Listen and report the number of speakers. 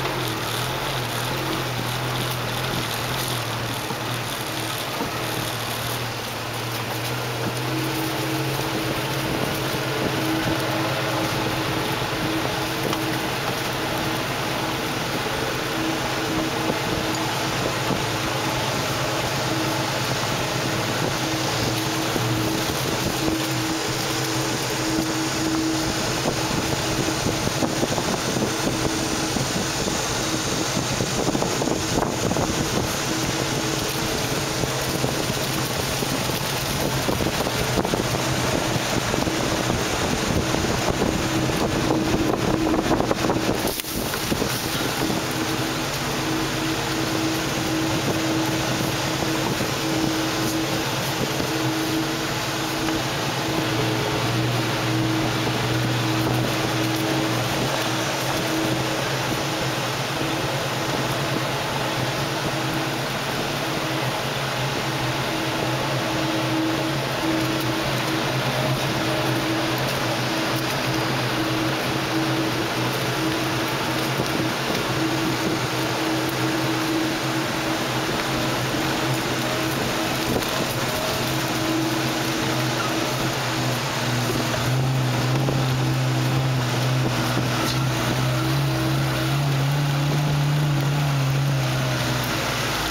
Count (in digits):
0